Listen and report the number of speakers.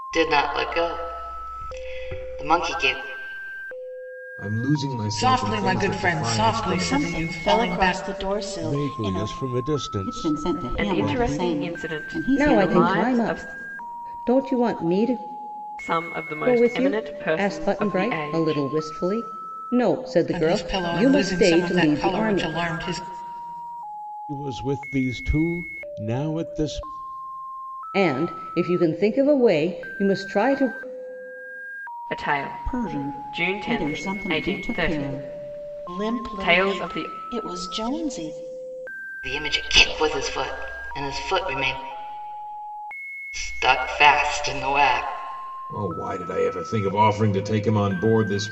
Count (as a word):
eight